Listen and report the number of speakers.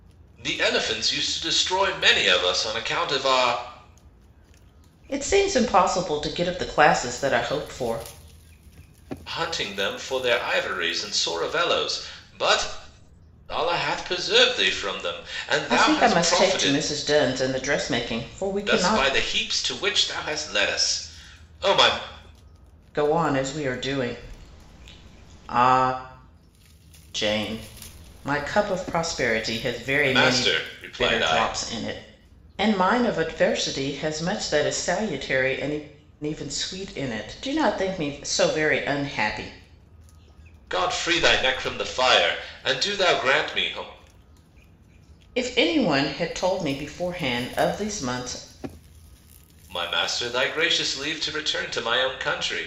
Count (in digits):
2